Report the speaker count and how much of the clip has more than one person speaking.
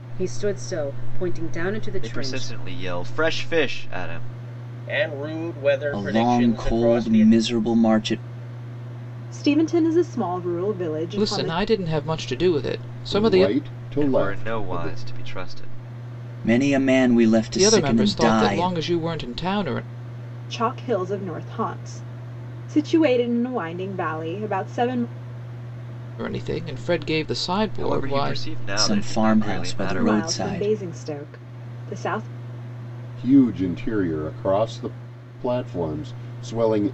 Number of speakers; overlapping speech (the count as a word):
seven, about 21%